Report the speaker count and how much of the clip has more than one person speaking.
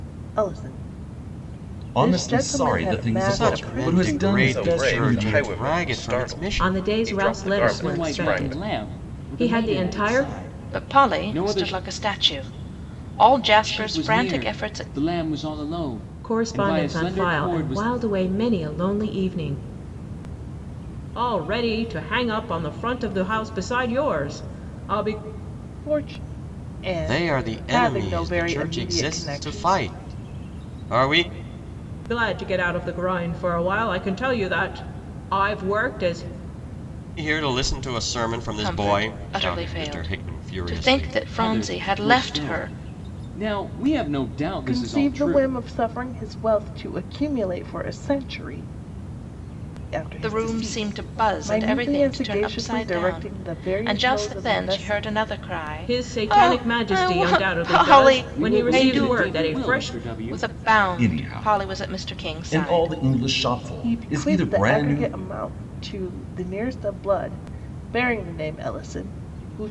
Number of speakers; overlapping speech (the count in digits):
7, about 48%